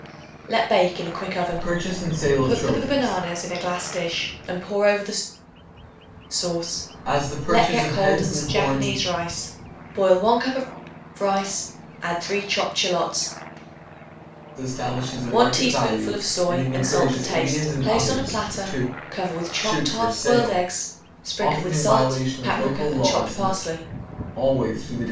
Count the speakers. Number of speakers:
2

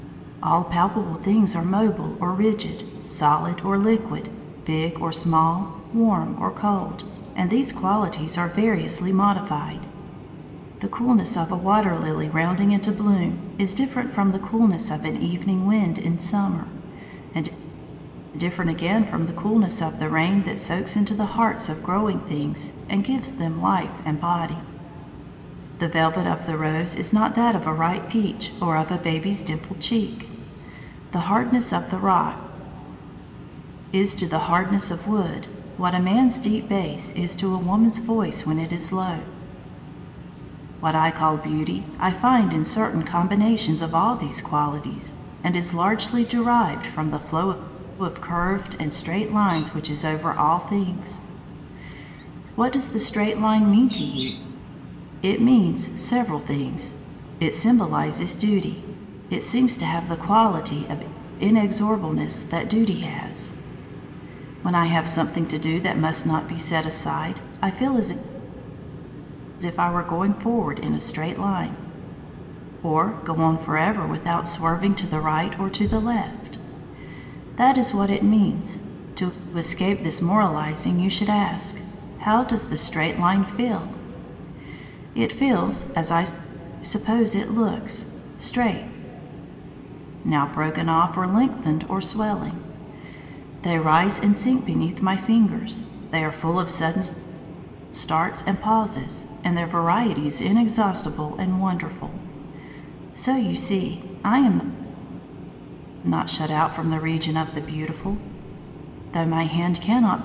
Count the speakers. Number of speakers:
1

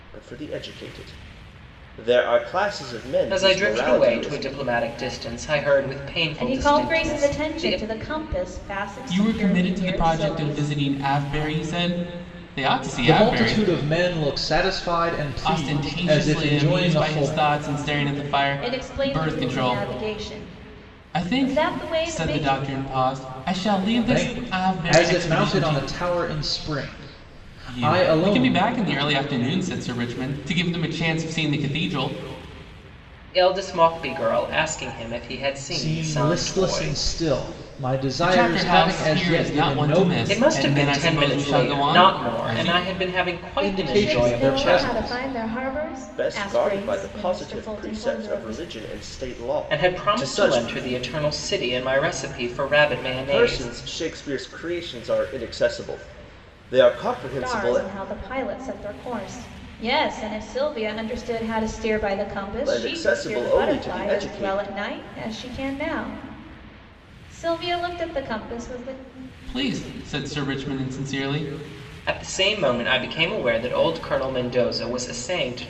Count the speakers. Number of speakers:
5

